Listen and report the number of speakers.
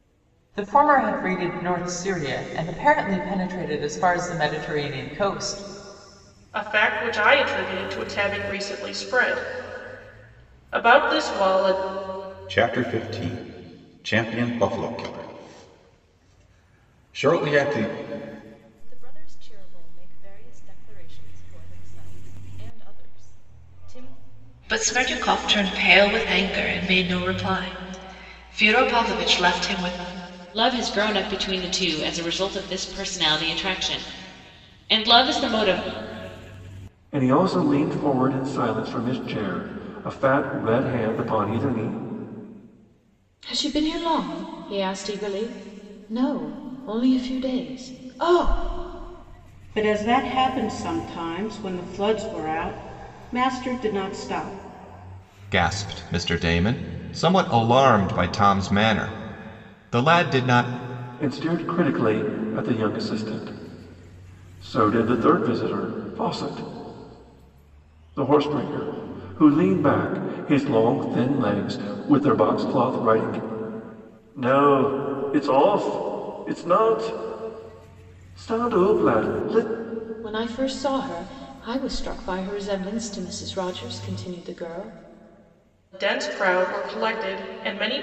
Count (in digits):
10